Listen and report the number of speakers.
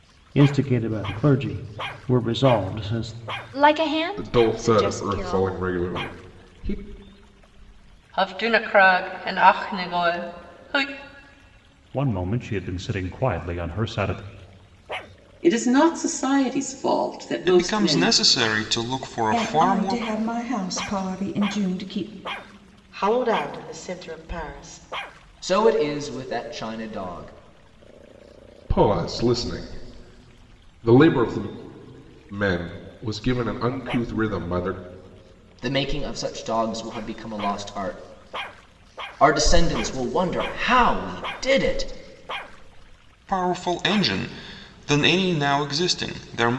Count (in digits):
10